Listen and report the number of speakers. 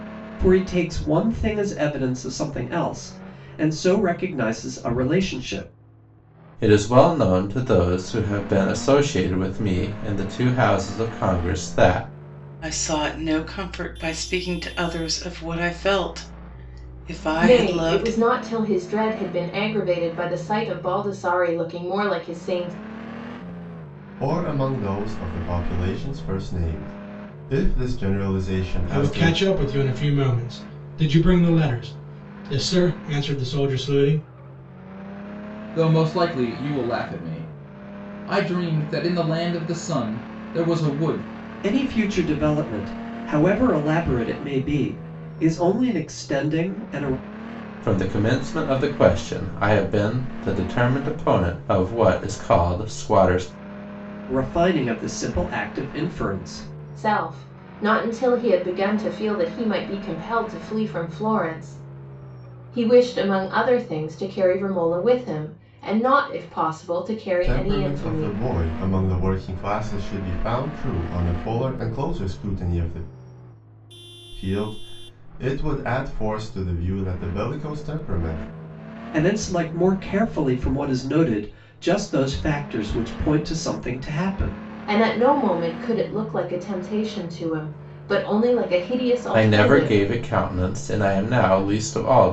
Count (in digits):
7